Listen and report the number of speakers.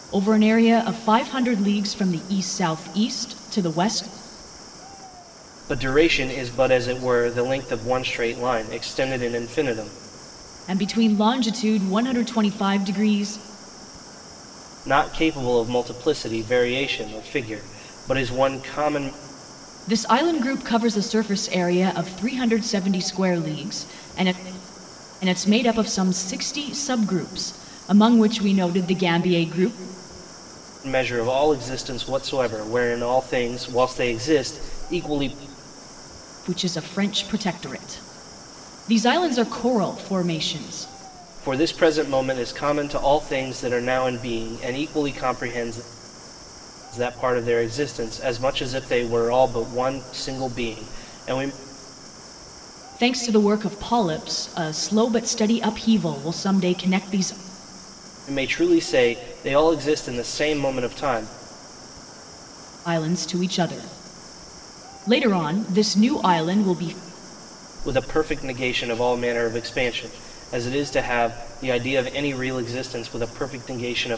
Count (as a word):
two